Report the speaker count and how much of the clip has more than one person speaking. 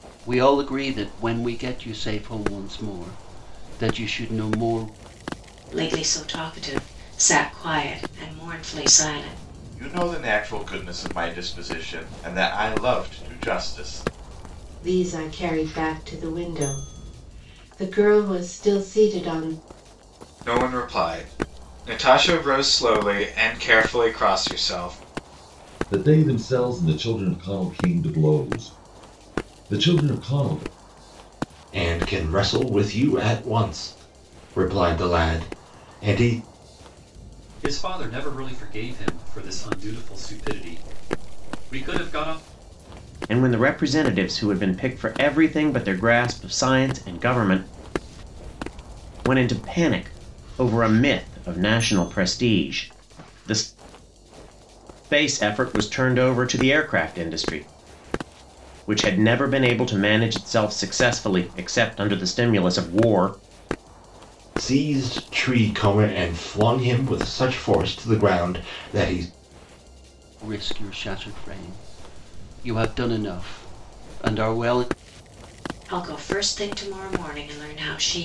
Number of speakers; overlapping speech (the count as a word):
nine, no overlap